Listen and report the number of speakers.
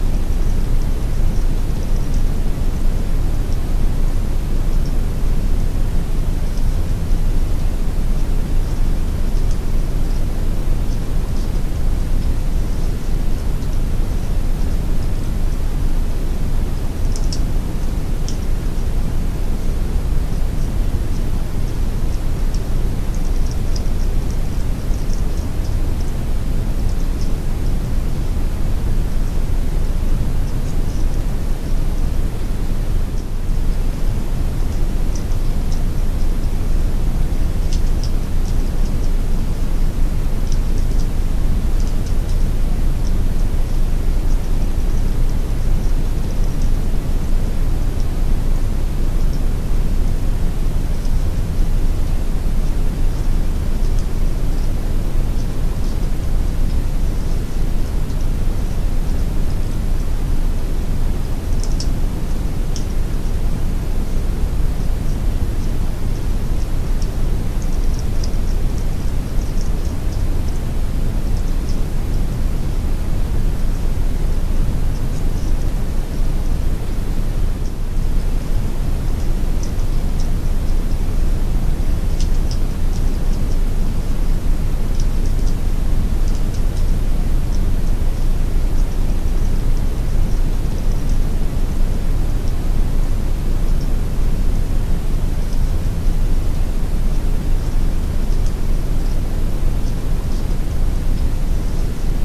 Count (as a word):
zero